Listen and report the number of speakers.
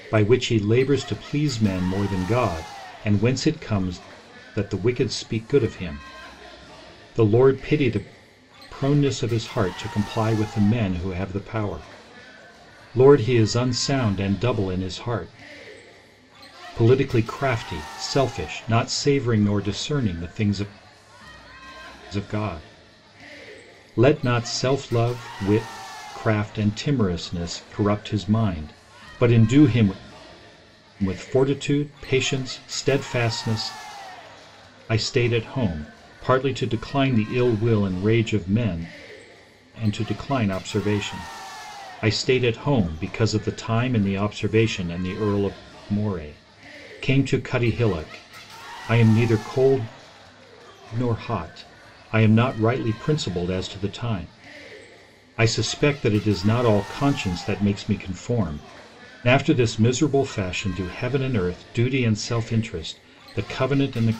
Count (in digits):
1